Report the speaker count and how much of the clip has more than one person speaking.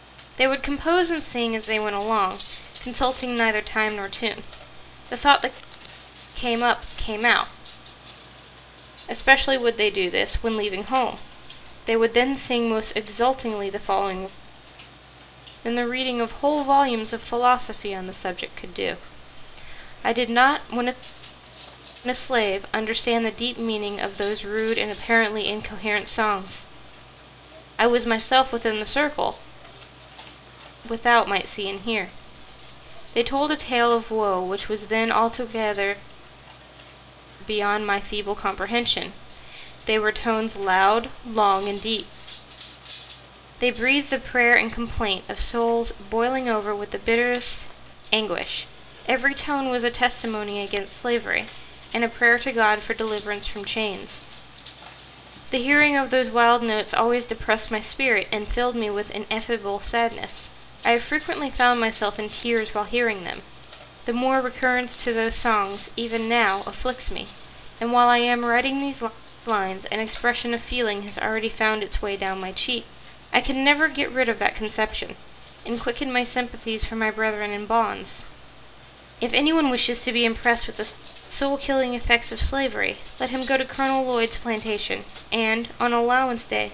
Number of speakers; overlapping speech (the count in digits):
1, no overlap